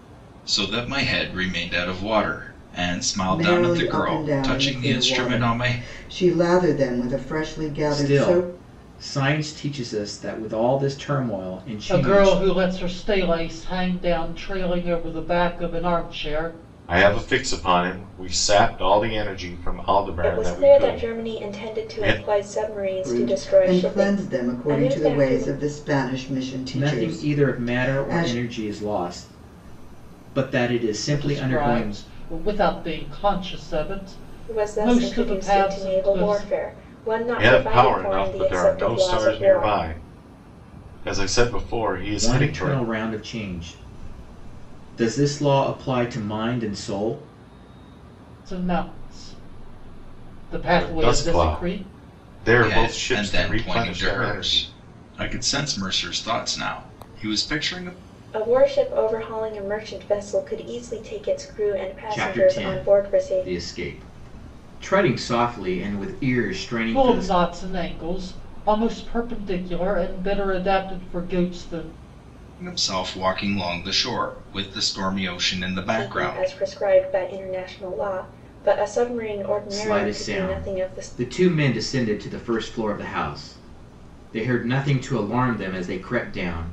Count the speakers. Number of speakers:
6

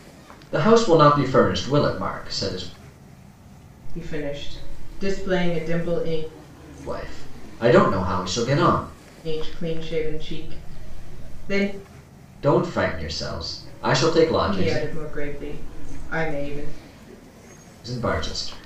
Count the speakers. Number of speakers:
2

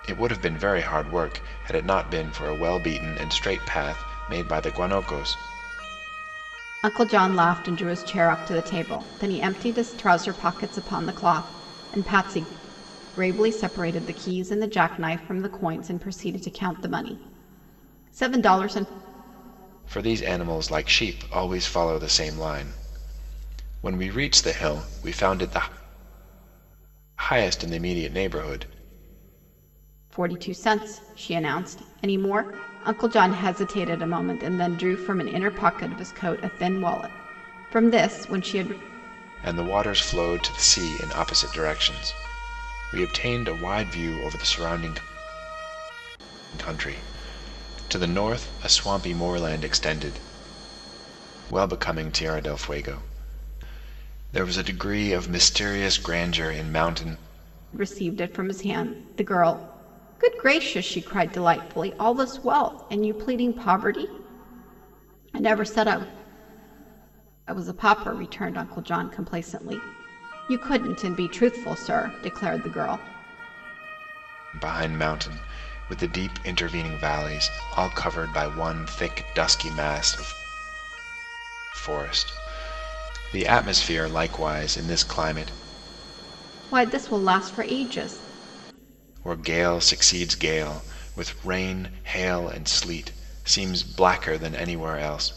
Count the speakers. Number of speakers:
2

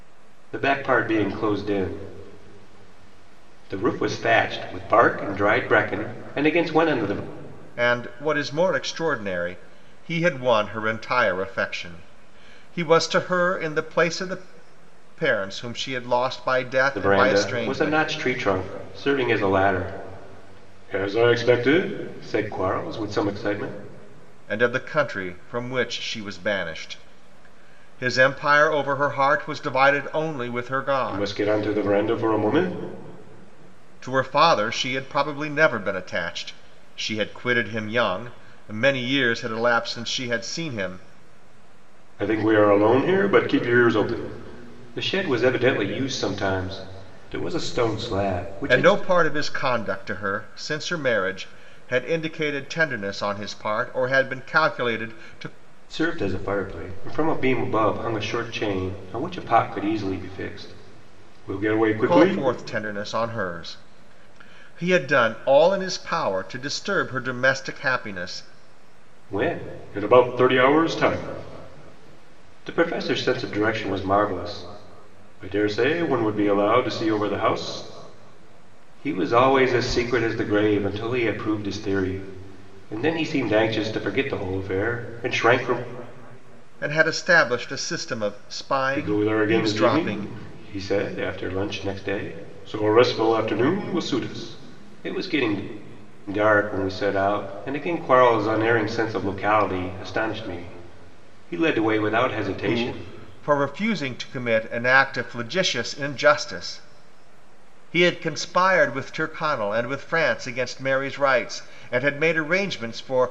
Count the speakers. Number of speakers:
2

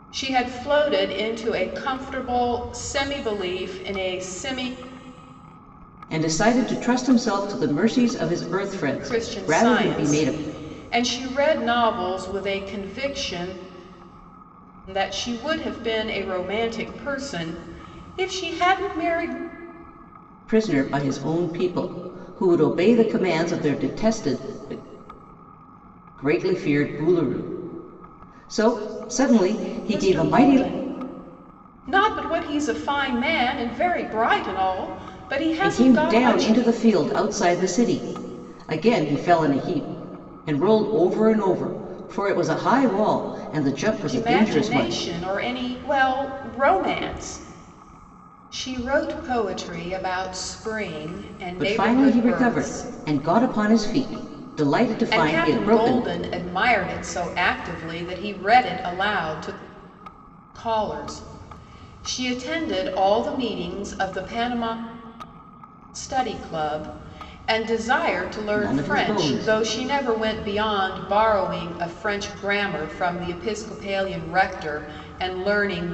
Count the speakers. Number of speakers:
2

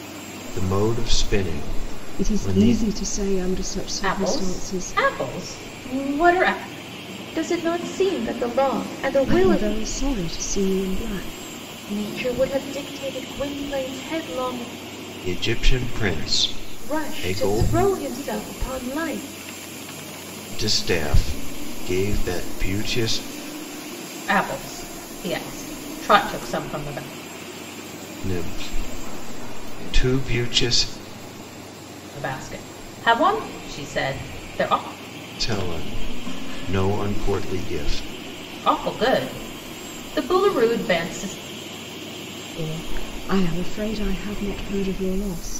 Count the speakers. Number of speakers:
4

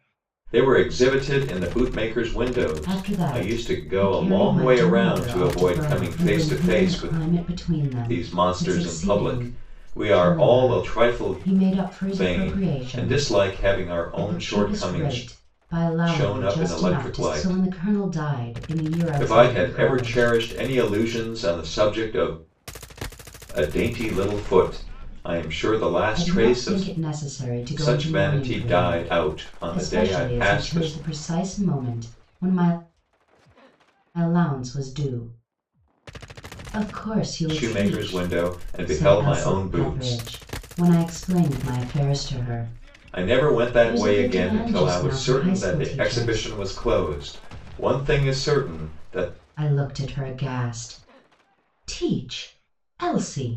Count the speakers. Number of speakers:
2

